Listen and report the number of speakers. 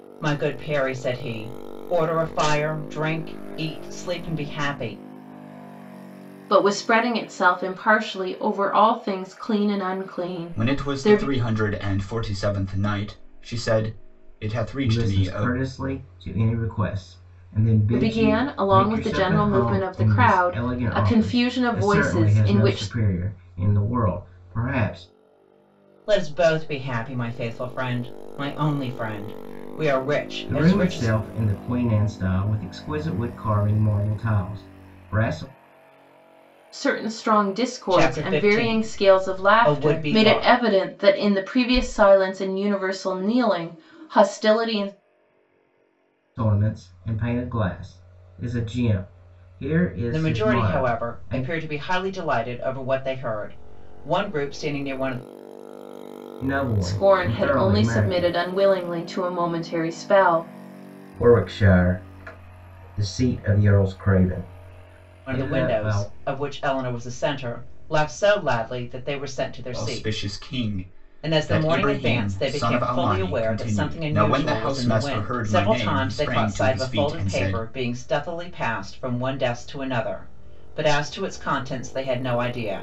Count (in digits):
4